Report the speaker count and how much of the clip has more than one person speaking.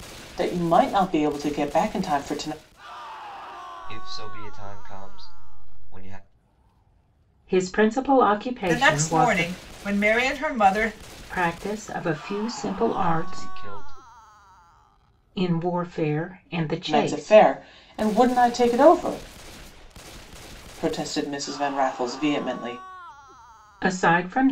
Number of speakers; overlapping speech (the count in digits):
4, about 8%